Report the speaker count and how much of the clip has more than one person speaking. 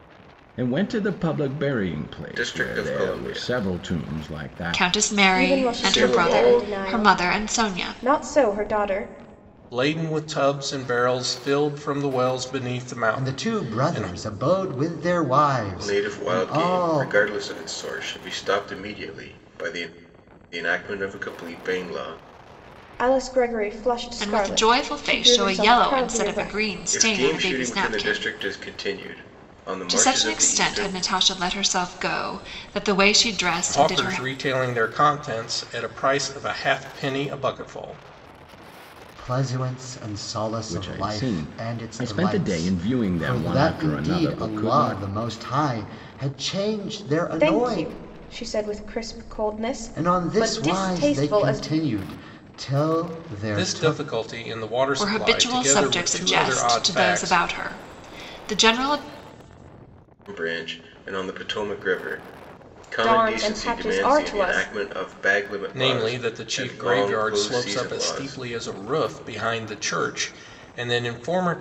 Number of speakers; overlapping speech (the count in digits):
6, about 39%